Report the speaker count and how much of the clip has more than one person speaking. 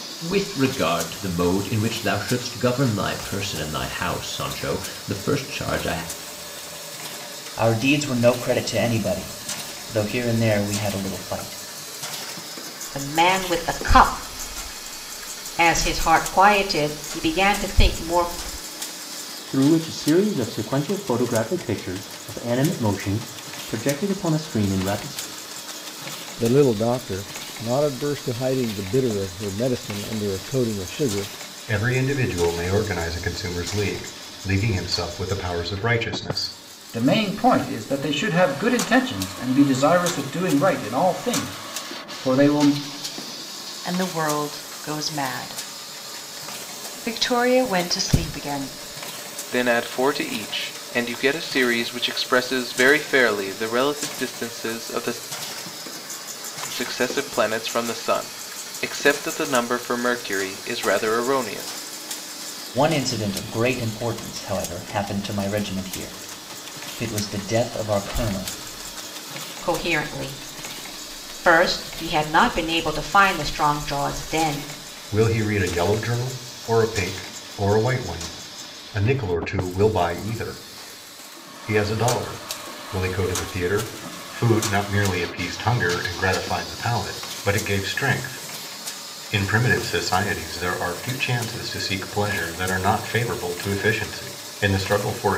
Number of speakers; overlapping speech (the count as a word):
nine, no overlap